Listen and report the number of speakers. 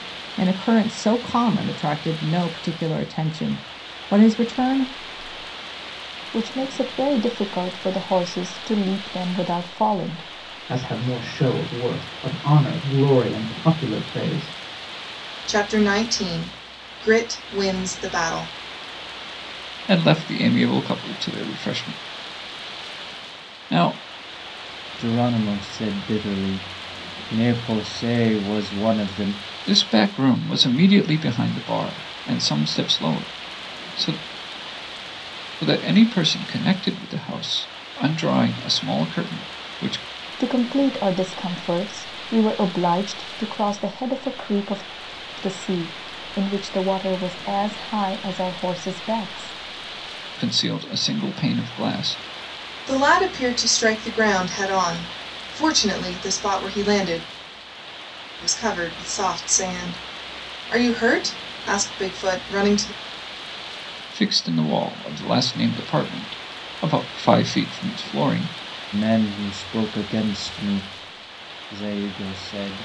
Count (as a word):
six